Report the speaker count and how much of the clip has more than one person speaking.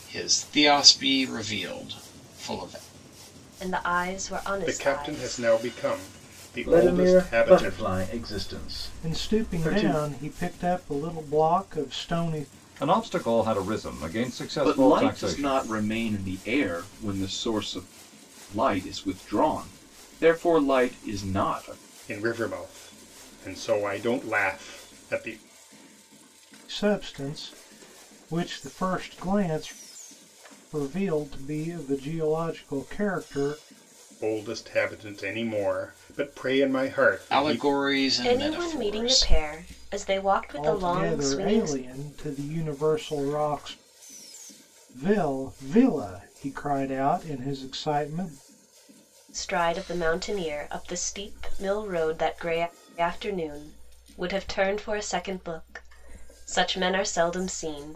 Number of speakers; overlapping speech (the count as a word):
seven, about 12%